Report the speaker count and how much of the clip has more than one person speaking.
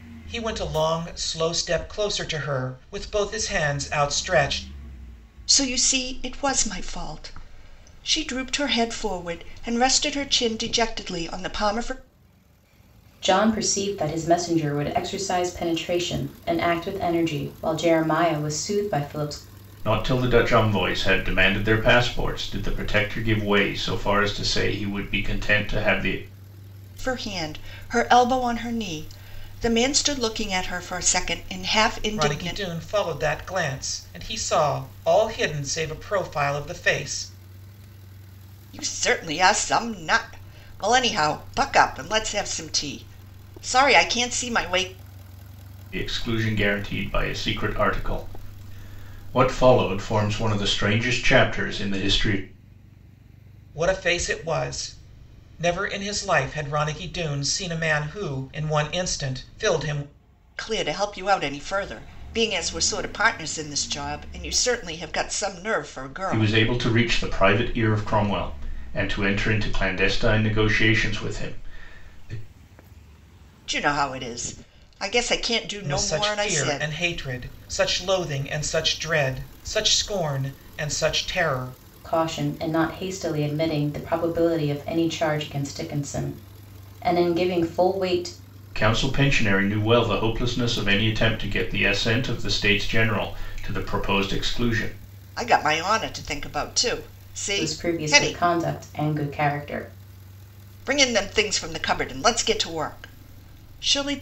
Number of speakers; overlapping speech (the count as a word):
four, about 3%